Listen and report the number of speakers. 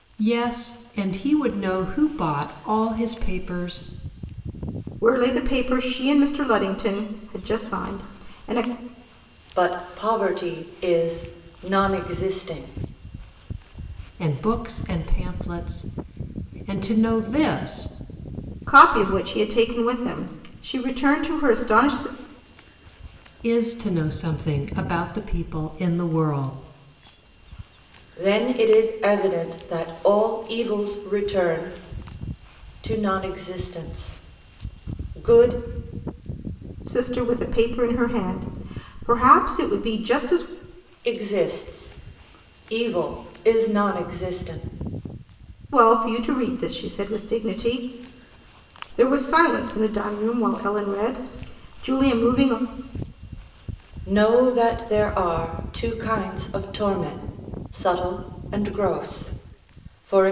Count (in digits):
3